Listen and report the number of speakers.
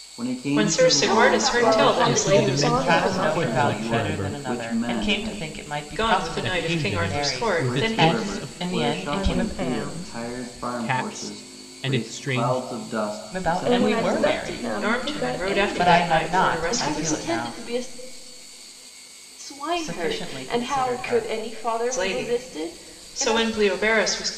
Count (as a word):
six